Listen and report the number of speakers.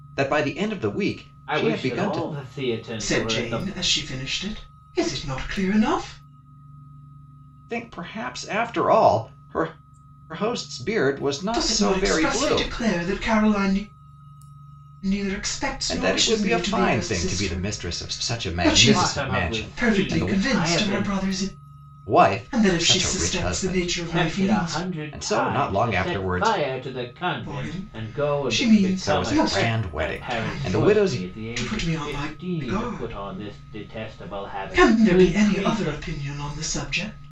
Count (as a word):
three